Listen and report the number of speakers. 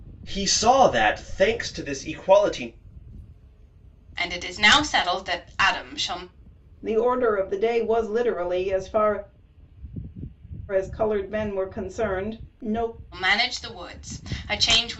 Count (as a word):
three